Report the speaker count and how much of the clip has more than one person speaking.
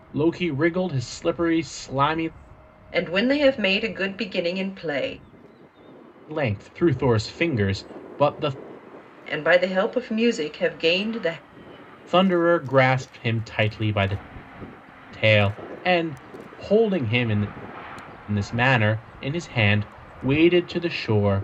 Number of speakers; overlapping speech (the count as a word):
two, no overlap